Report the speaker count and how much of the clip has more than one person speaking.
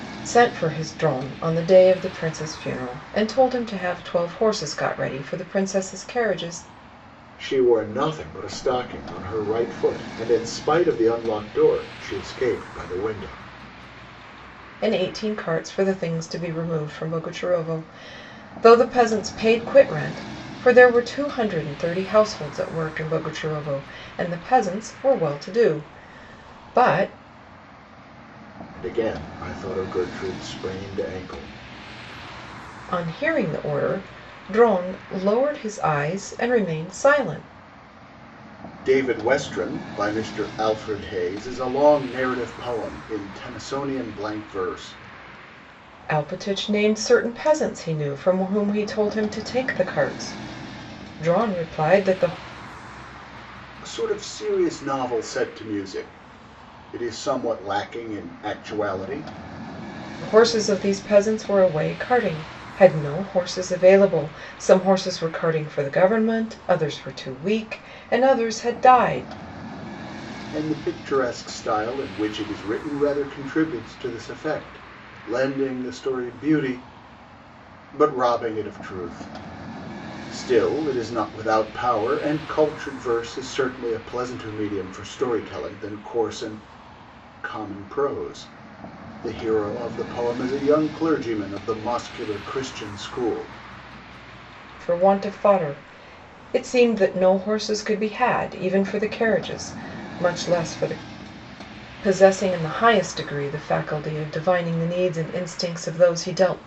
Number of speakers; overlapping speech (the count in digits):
2, no overlap